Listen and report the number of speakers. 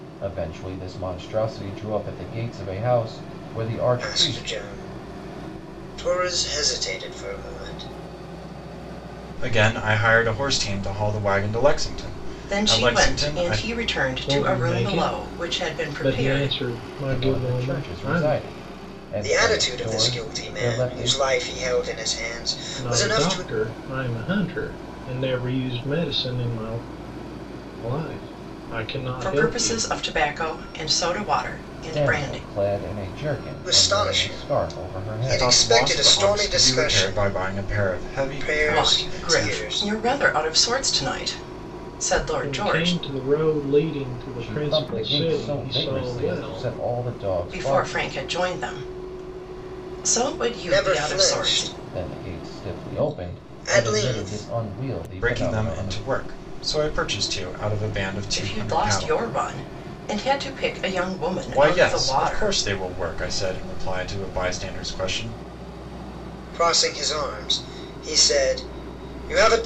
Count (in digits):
5